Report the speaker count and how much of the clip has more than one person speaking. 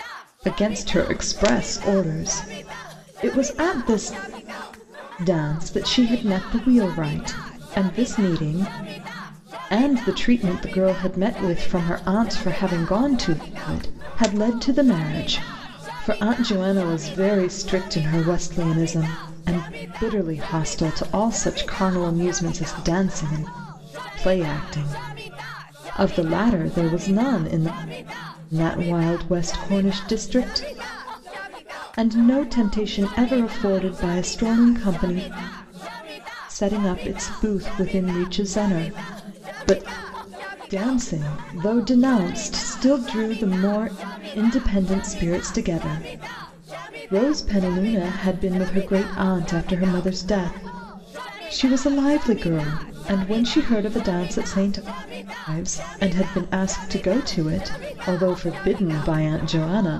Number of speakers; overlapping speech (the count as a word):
one, no overlap